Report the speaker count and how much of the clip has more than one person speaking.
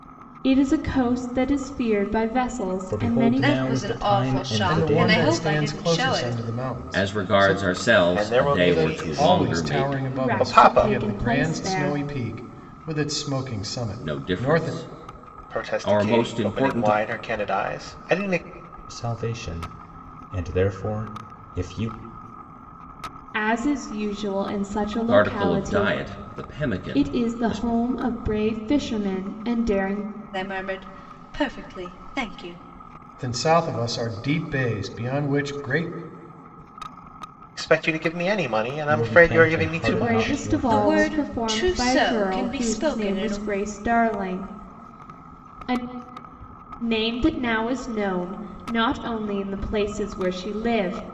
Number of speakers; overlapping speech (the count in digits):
6, about 33%